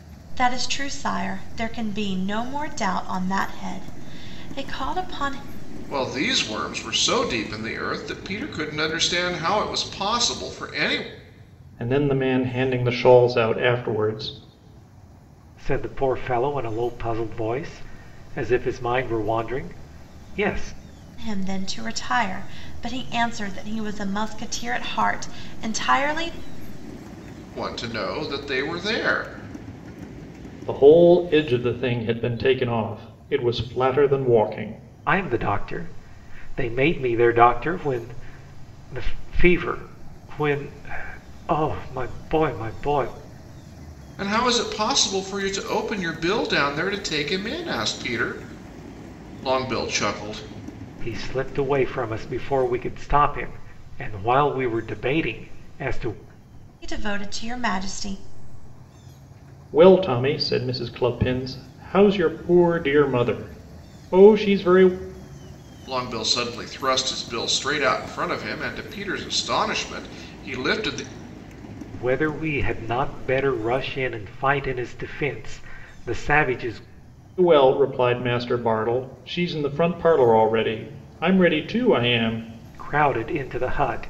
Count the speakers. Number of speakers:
four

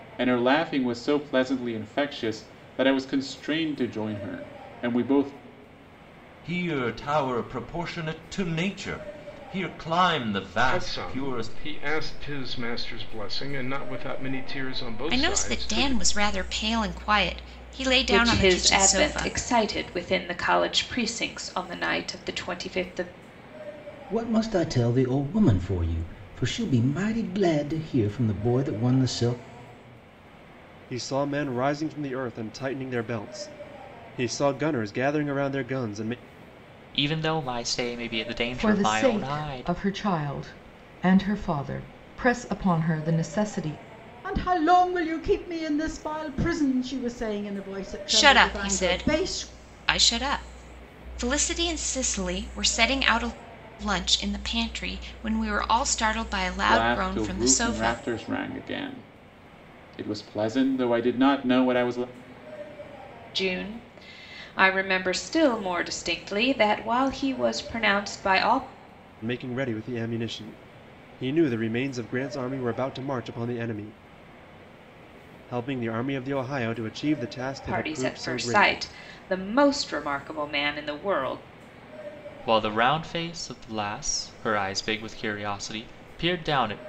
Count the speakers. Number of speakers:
ten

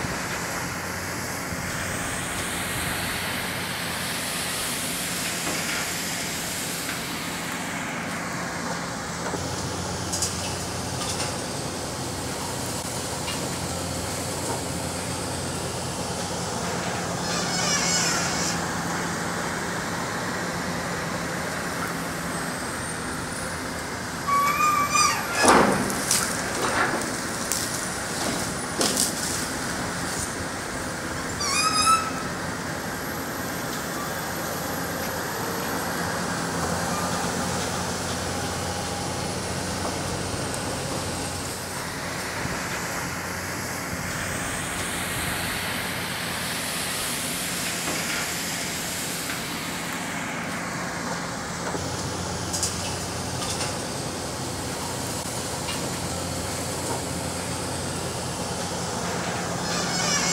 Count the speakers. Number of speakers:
zero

